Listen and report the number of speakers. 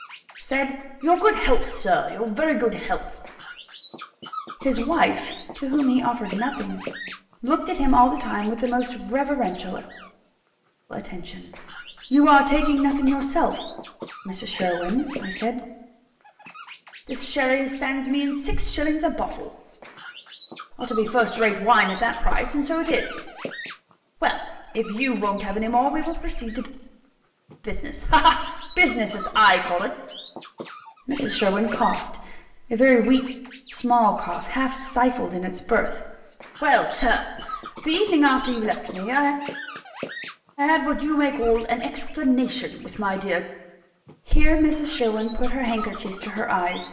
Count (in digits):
1